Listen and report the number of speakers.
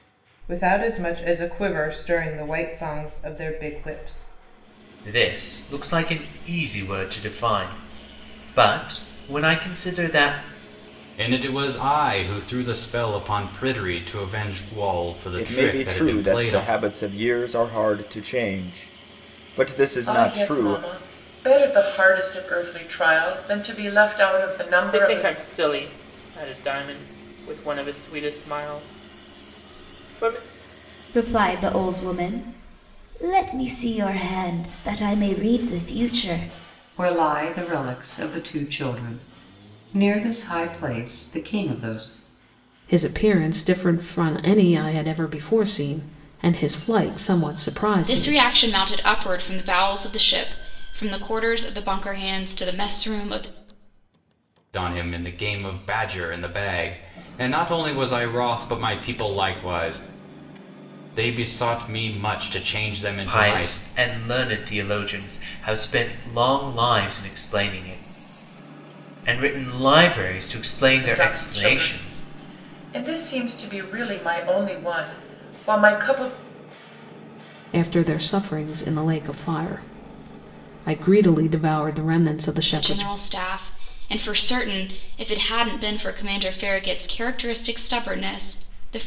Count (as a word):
ten